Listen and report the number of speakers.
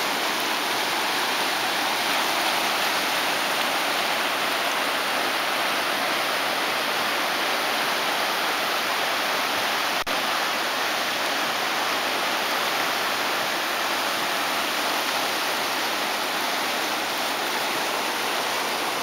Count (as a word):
zero